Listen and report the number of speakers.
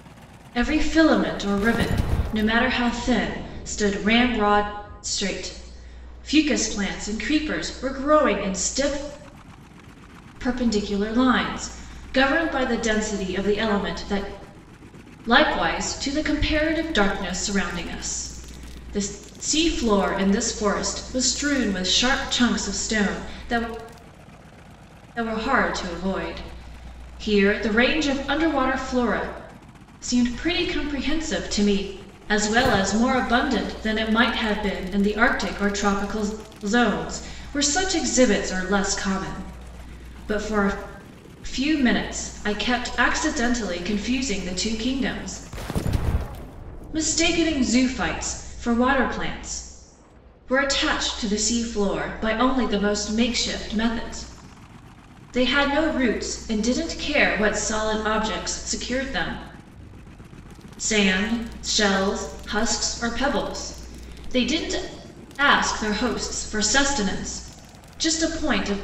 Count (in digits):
1